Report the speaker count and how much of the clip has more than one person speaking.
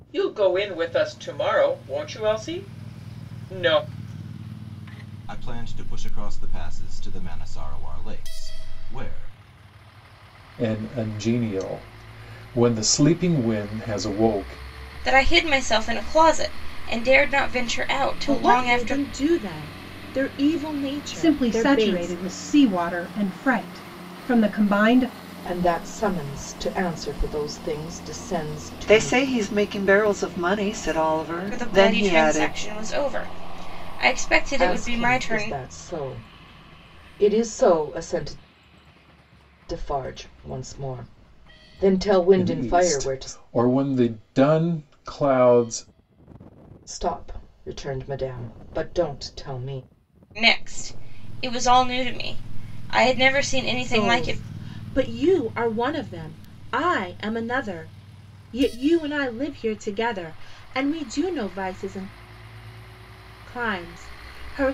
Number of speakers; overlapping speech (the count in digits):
8, about 9%